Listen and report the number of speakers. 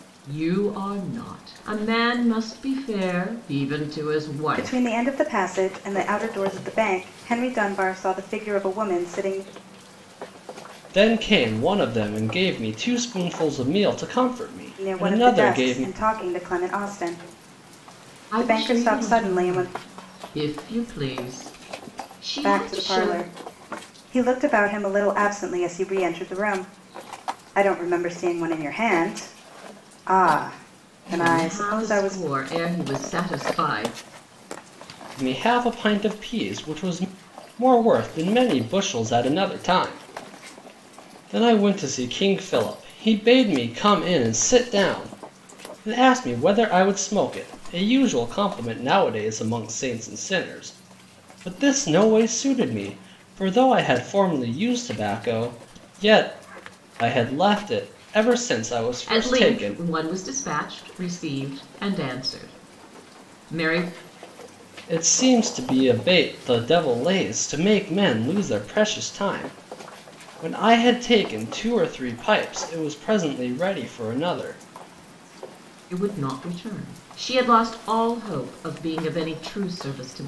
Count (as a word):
three